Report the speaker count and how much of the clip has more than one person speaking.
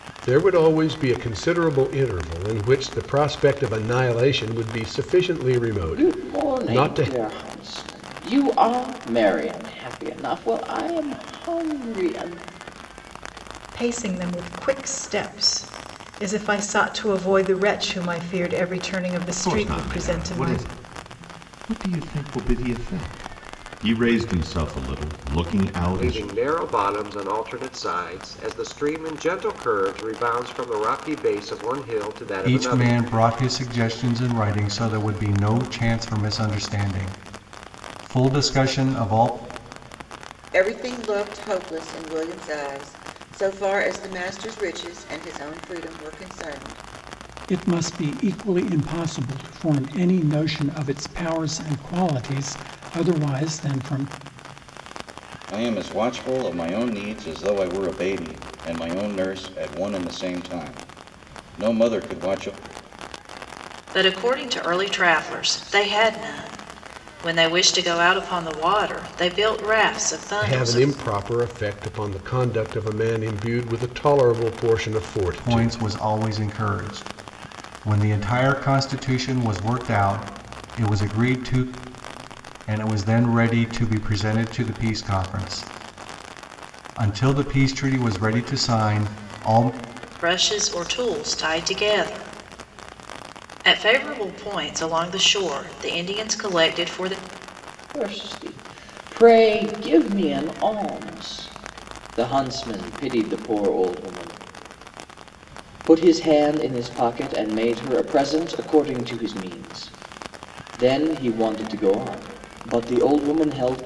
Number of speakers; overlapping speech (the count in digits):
10, about 4%